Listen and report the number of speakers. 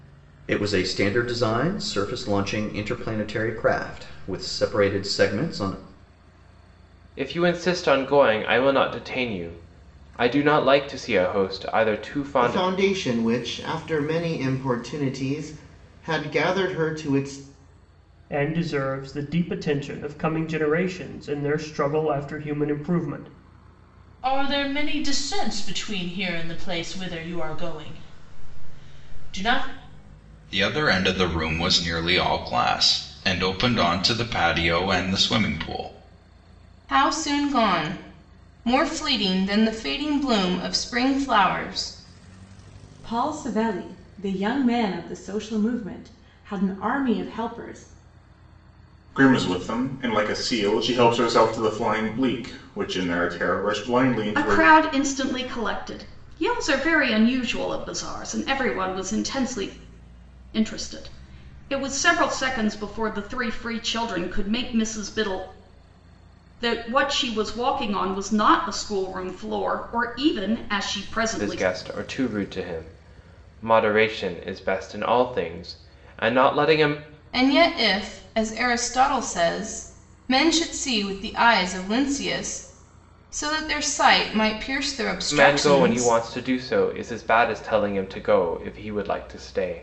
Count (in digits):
10